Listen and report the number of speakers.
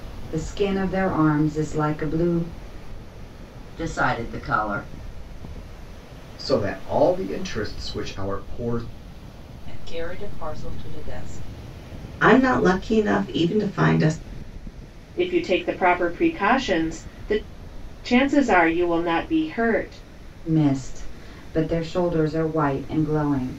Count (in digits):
6